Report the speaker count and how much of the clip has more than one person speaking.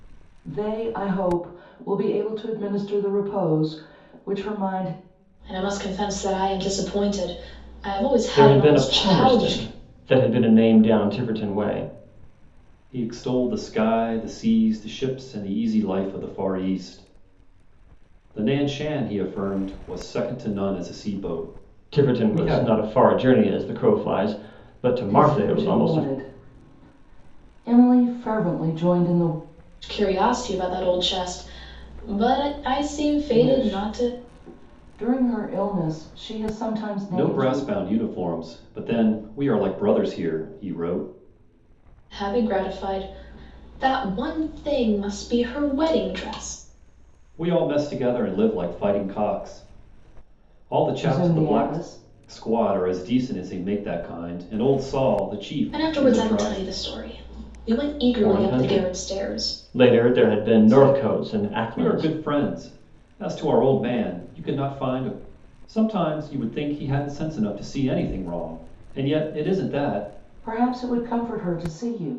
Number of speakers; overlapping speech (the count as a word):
four, about 13%